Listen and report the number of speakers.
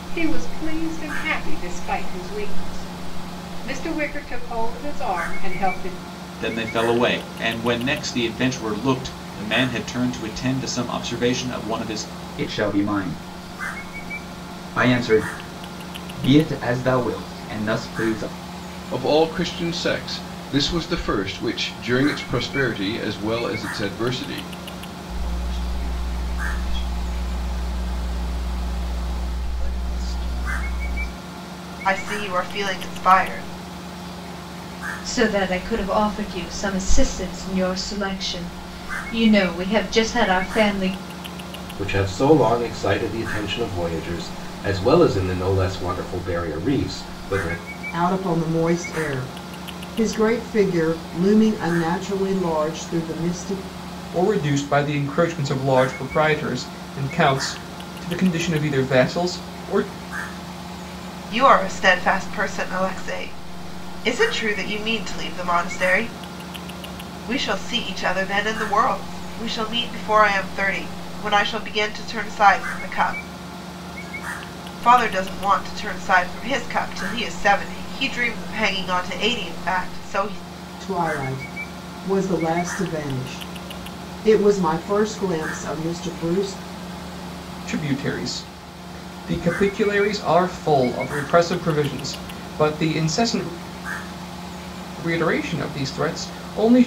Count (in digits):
10